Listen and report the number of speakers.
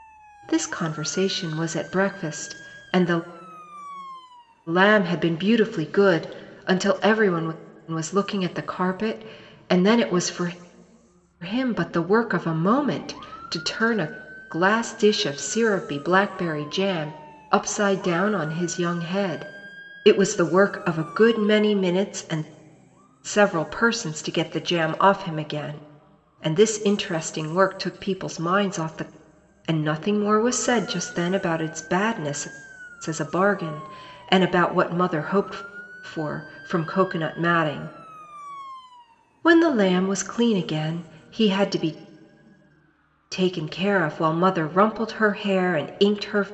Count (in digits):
1